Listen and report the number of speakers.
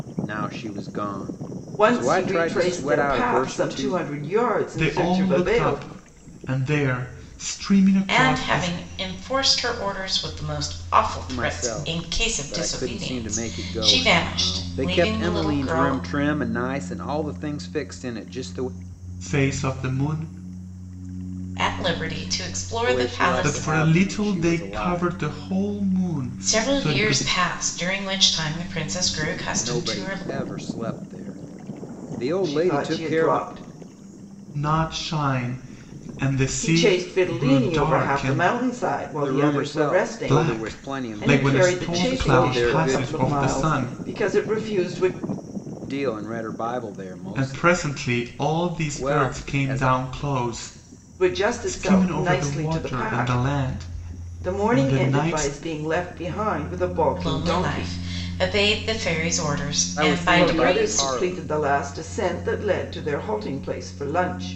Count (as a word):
four